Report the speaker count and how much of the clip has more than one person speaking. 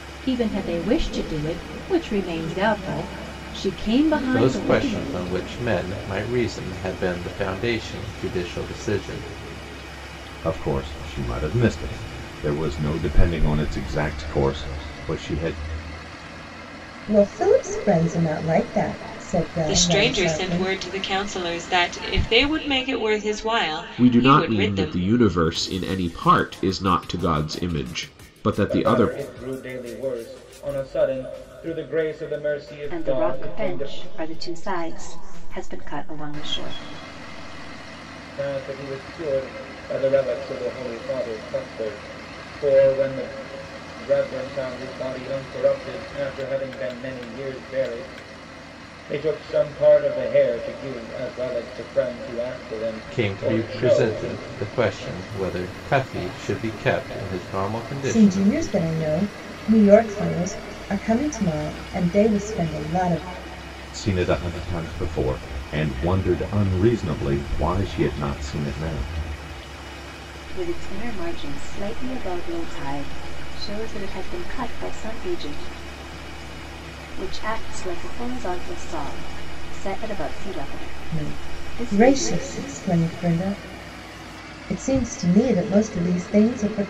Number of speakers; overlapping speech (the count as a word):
eight, about 9%